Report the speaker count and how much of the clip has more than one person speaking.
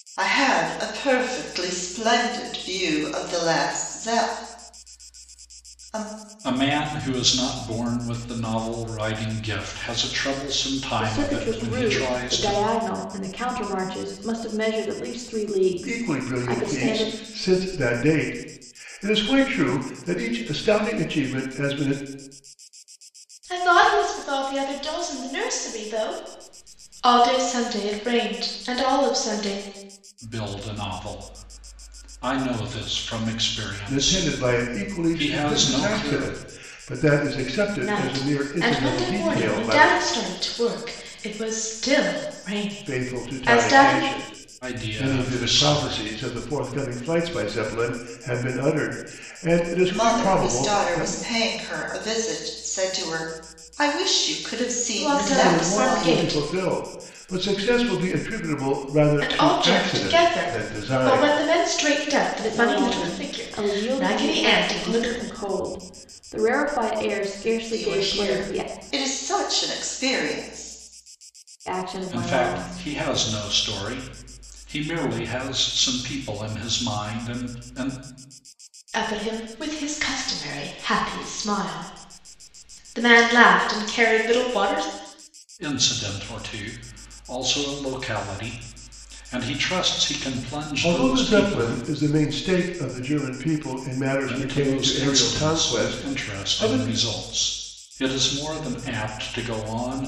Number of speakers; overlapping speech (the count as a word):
five, about 23%